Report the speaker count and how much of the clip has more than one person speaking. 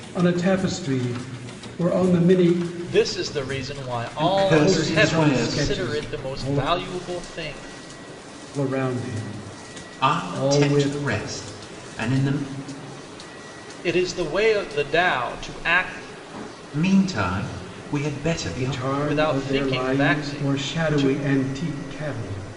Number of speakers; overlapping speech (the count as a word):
three, about 28%